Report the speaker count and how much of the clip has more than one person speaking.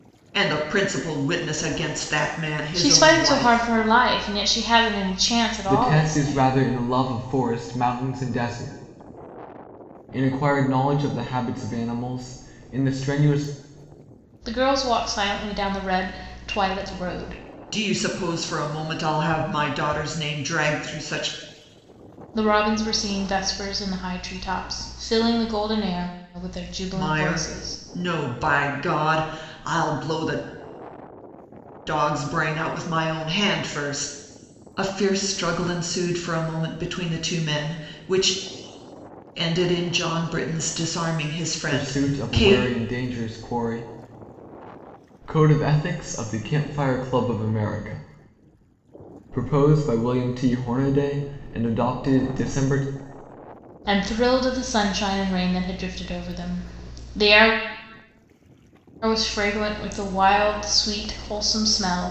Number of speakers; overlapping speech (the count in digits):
3, about 6%